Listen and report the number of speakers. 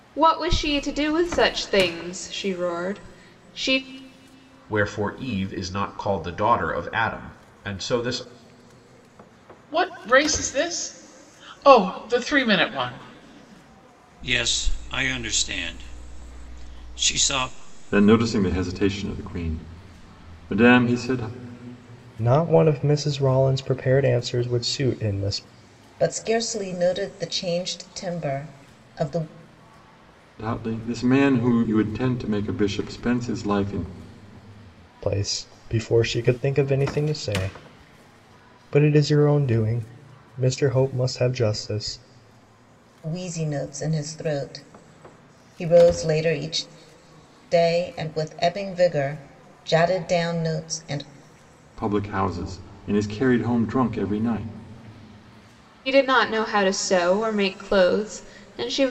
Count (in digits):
7